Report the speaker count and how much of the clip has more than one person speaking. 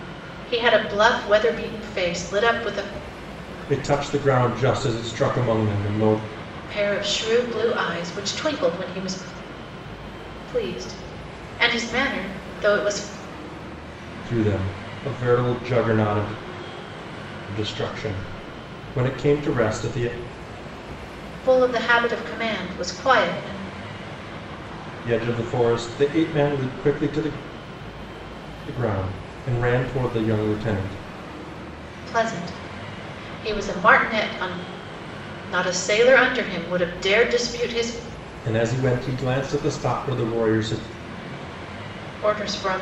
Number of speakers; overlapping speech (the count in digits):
2, no overlap